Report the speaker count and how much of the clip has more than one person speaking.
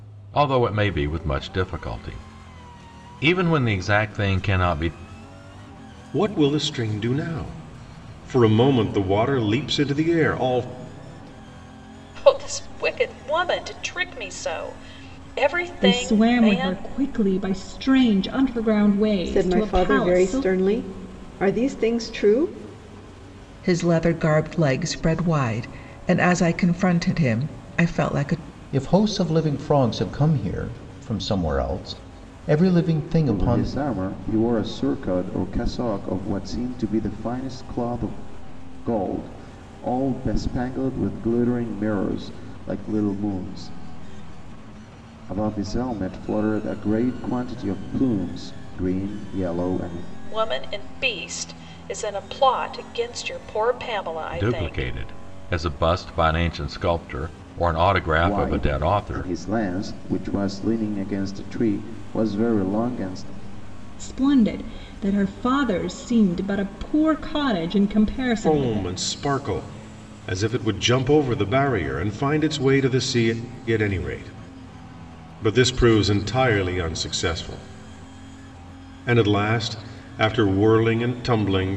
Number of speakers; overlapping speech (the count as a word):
eight, about 6%